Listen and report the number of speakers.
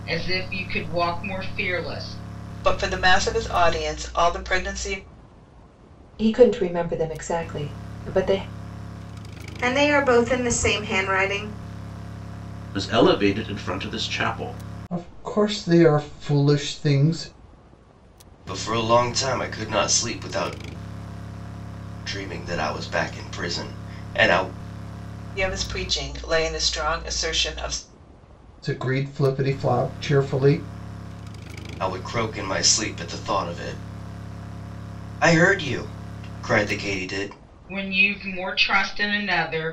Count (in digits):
7